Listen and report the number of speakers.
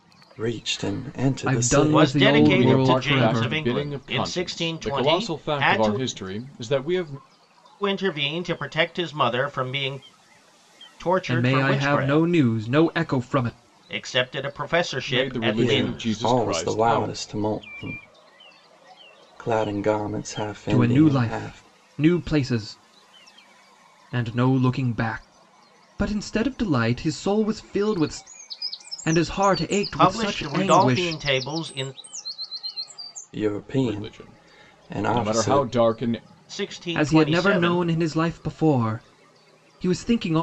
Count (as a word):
four